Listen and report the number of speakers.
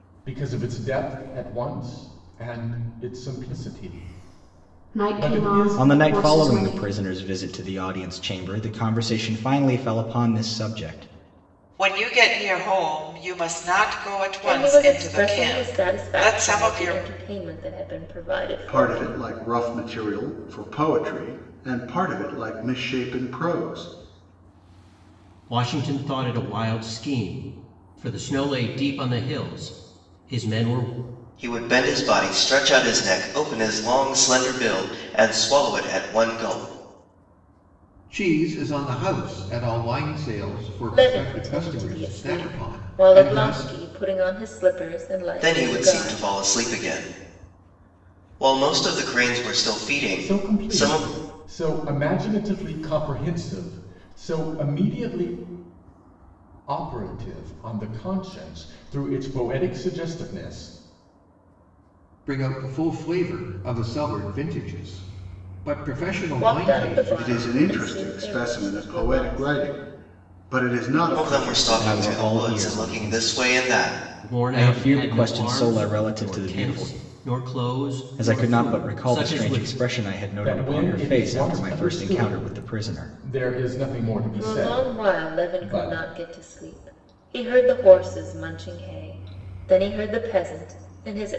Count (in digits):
9